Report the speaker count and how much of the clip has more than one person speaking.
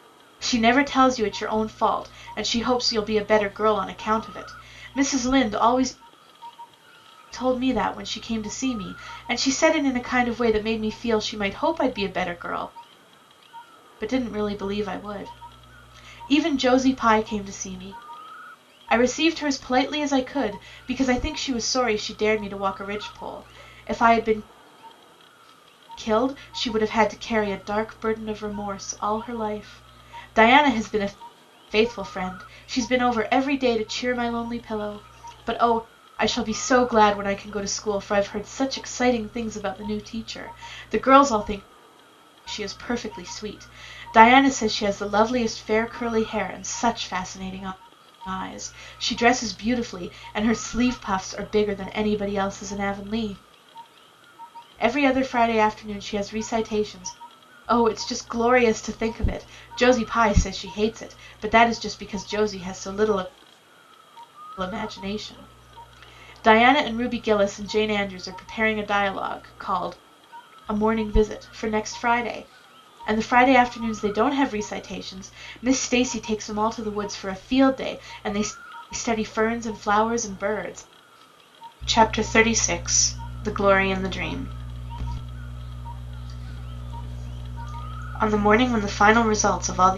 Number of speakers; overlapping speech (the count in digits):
1, no overlap